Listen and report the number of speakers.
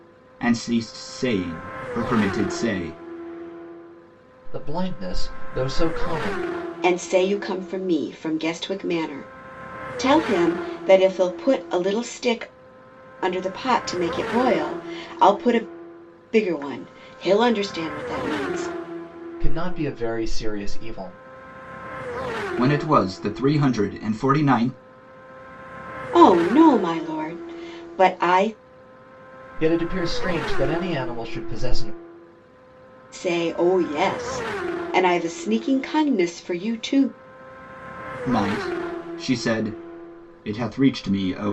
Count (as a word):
three